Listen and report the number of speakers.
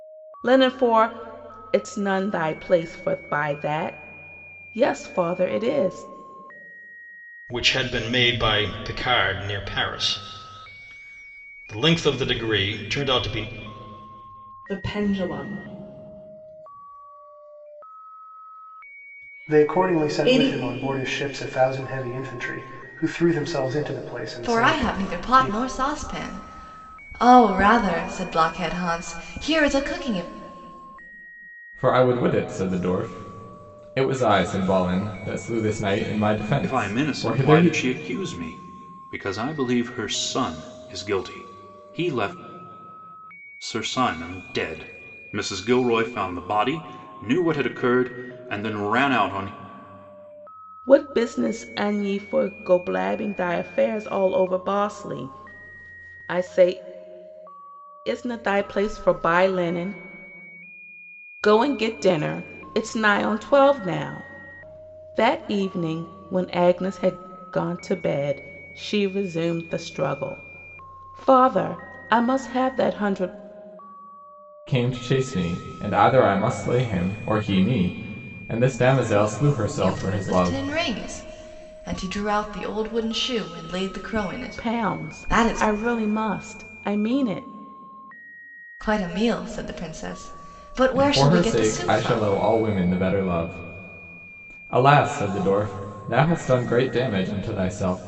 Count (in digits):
7